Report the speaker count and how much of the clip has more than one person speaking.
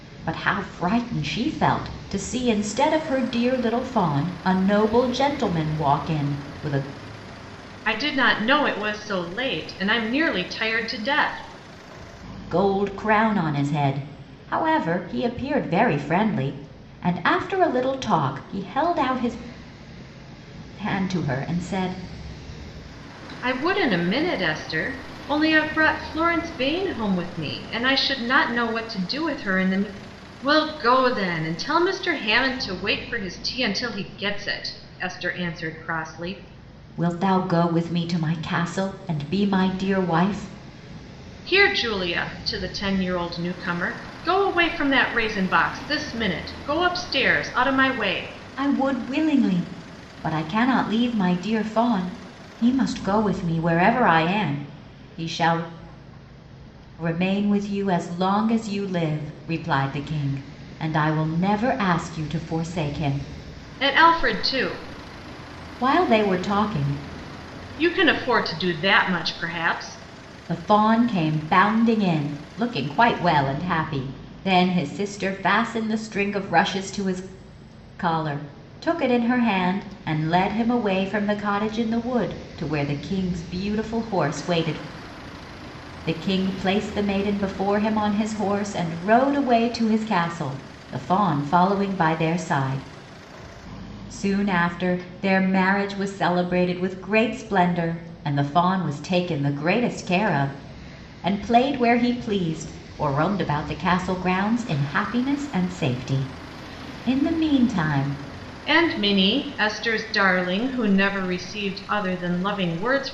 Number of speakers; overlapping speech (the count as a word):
two, no overlap